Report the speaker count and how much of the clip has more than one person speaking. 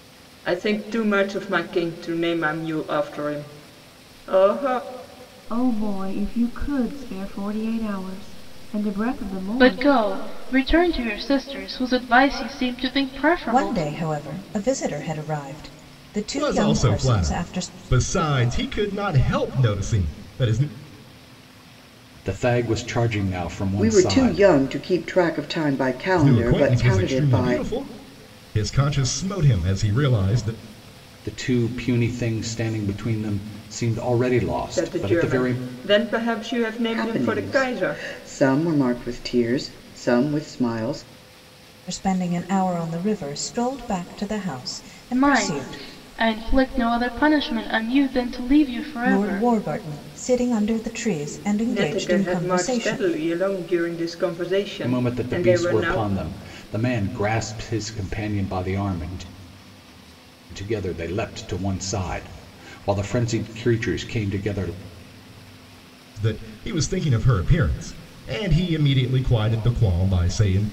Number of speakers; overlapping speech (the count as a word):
seven, about 15%